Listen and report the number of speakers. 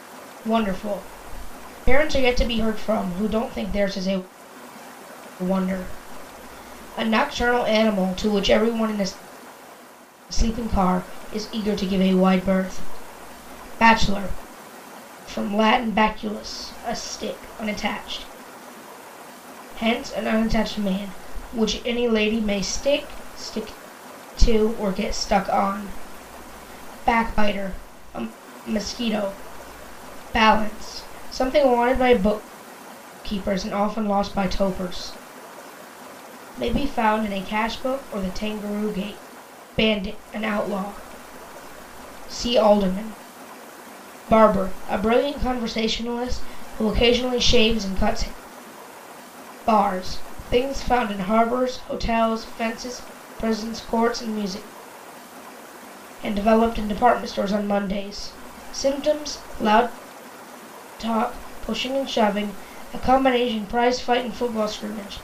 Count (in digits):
1